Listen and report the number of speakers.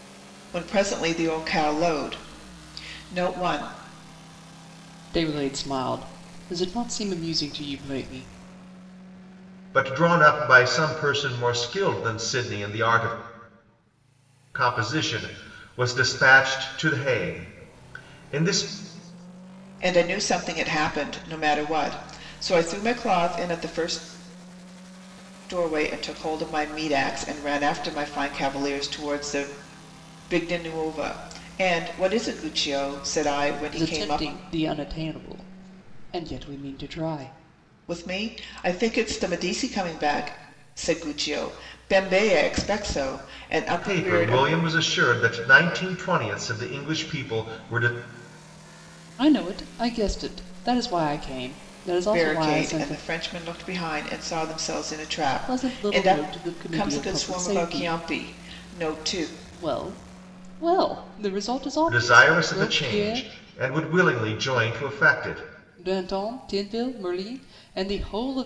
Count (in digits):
3